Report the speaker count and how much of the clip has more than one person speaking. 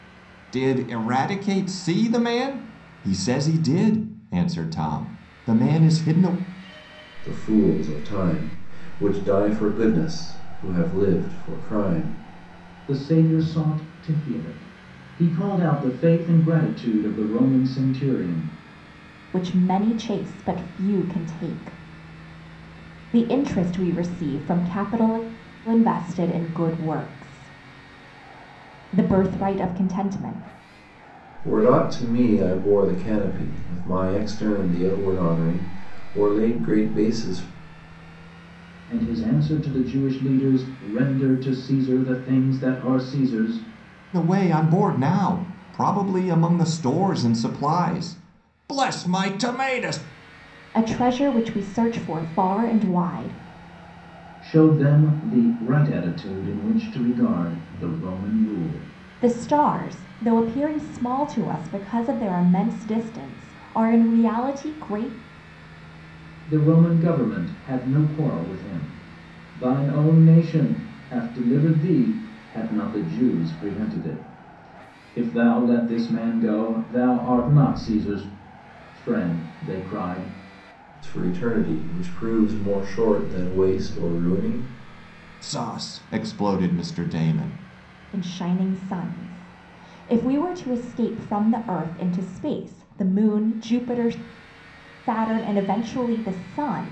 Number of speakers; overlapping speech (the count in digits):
4, no overlap